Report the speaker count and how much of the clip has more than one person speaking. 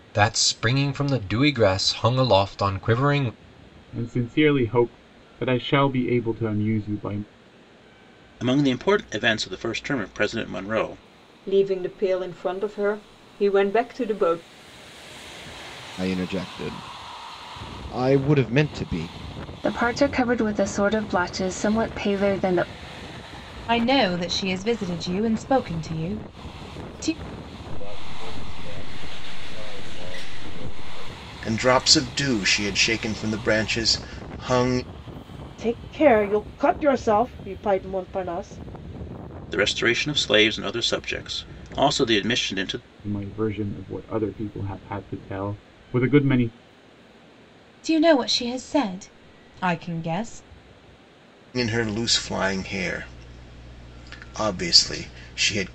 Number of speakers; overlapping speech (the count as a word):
ten, no overlap